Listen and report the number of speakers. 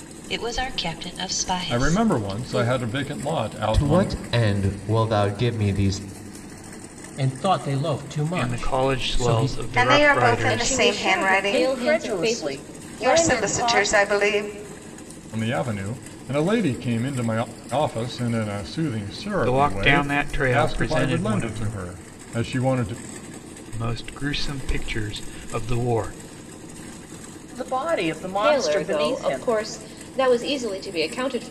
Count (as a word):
eight